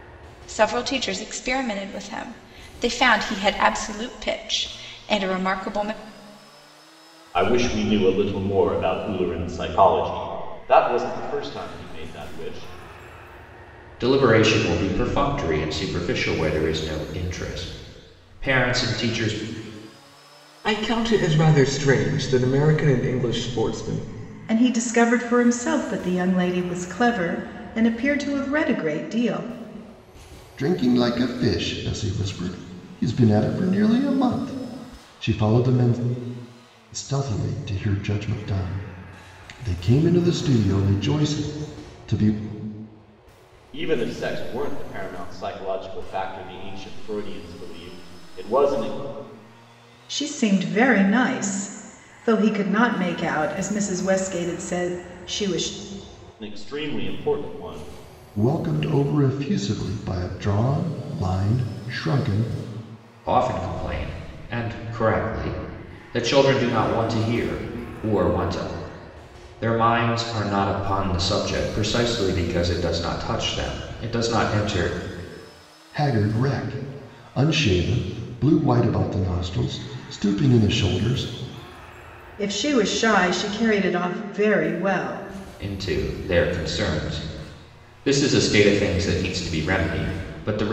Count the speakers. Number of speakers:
6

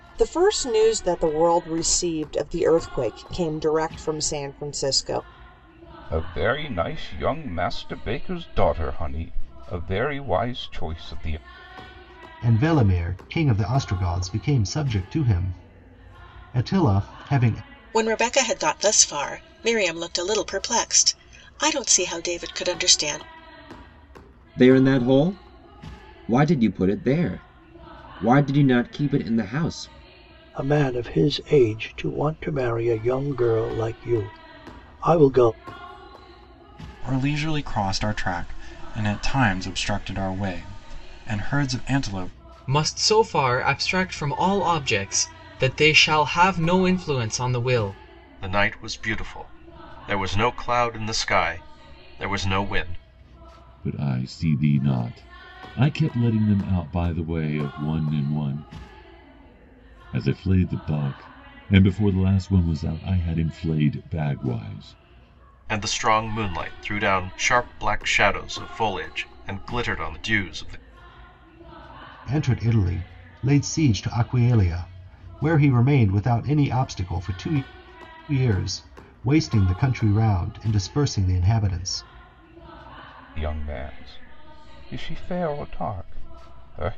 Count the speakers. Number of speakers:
10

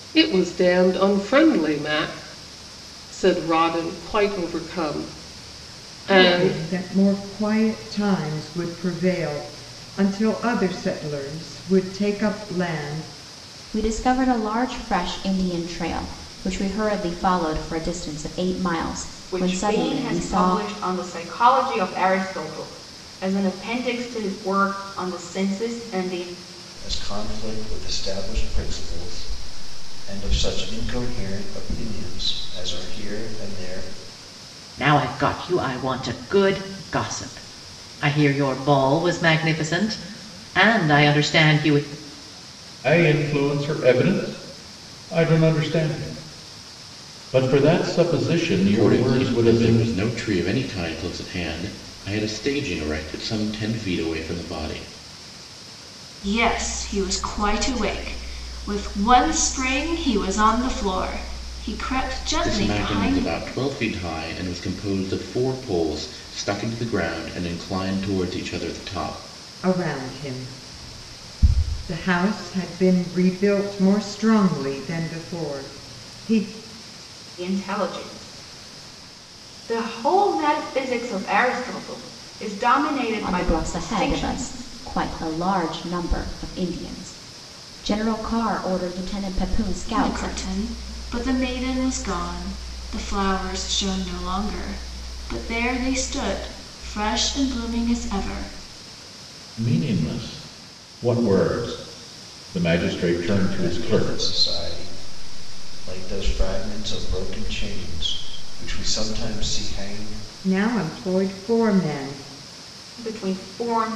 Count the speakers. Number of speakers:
9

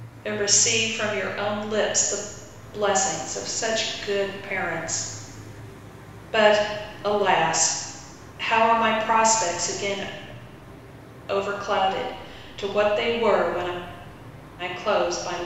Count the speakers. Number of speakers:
1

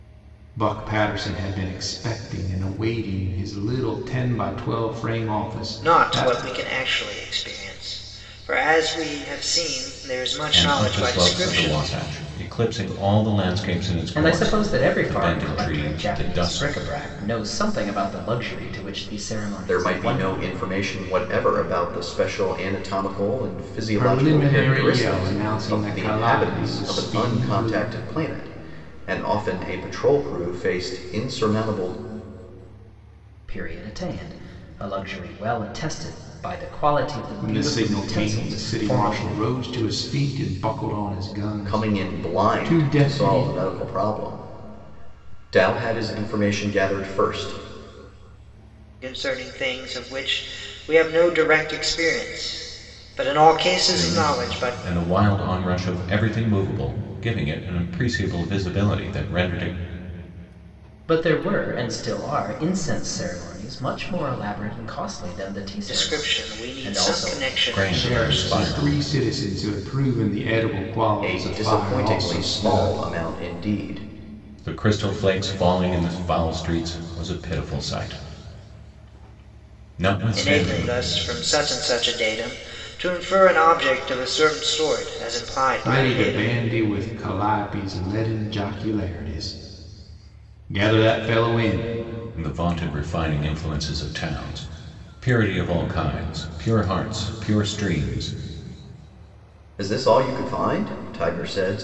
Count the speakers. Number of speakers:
5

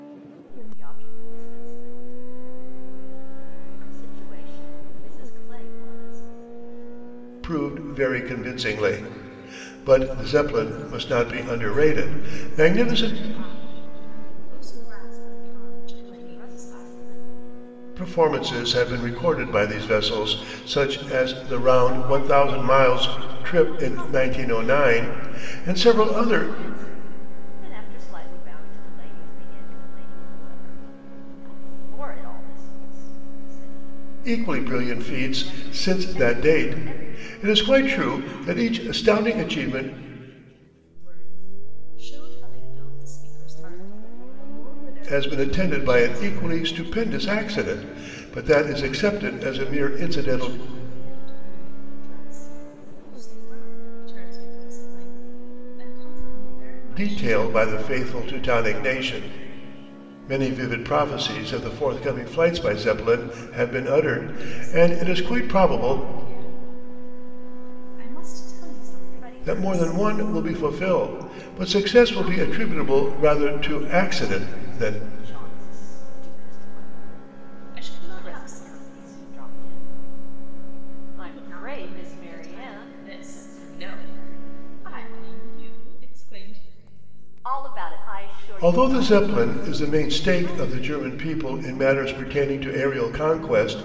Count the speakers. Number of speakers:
3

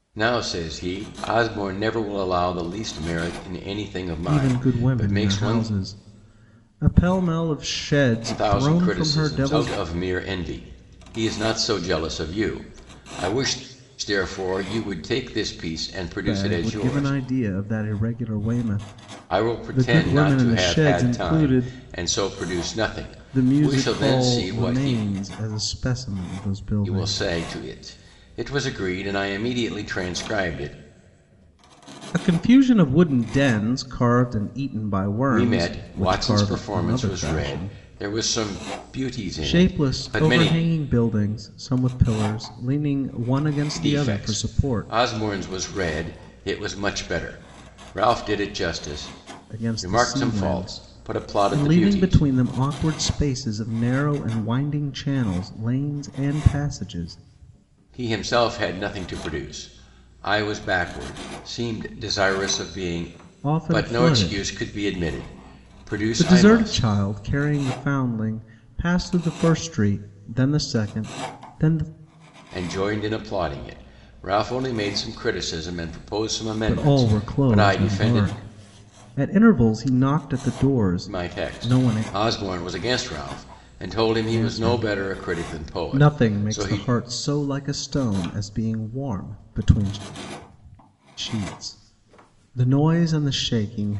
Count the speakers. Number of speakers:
2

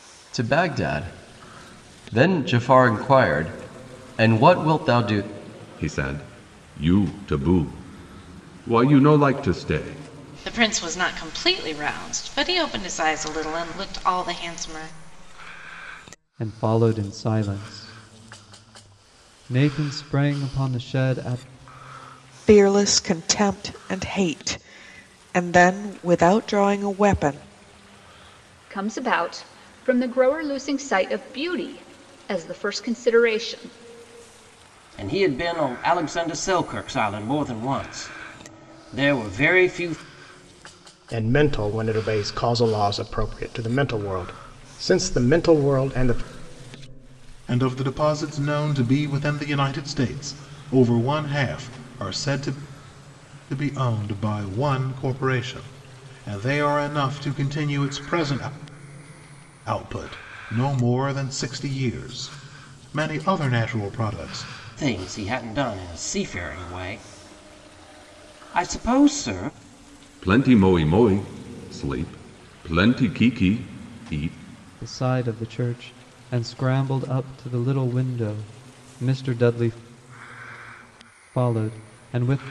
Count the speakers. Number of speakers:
9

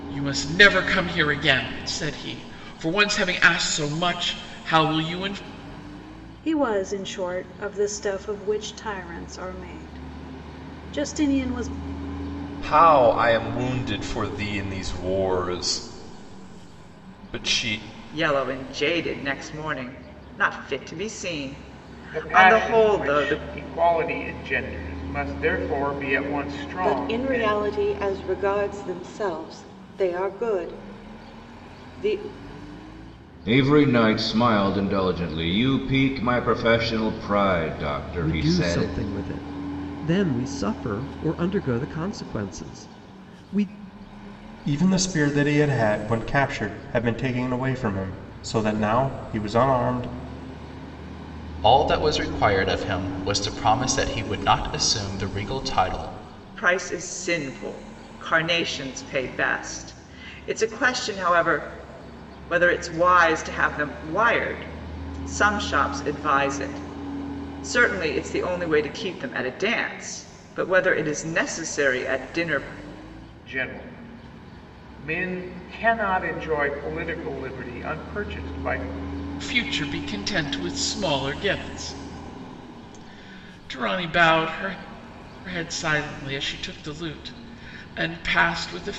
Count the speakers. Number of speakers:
10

